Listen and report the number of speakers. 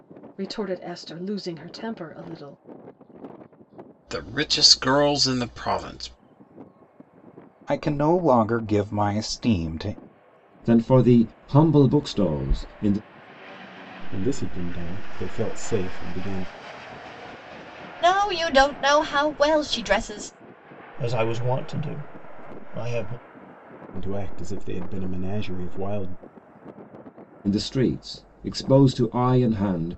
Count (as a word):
seven